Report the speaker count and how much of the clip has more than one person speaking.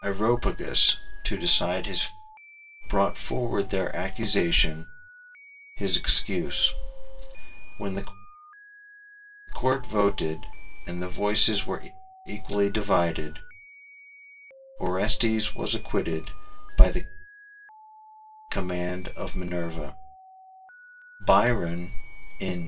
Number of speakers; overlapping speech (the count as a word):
one, no overlap